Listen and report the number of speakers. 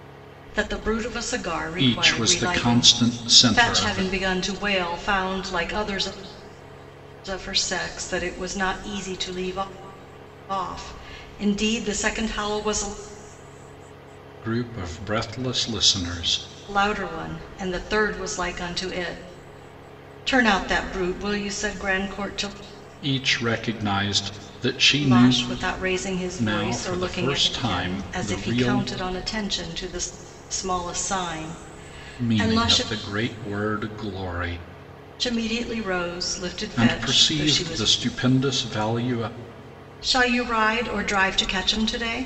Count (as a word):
two